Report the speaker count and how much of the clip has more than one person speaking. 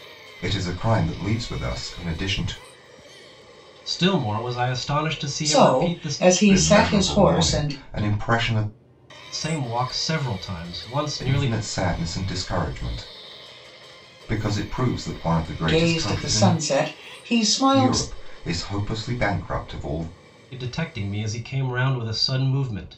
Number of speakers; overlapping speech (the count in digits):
3, about 16%